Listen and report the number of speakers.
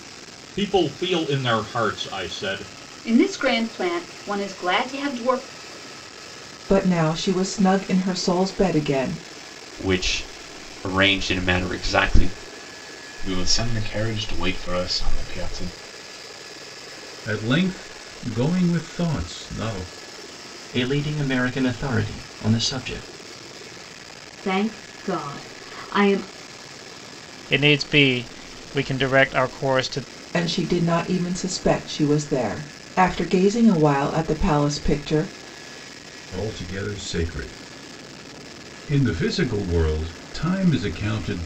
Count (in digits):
9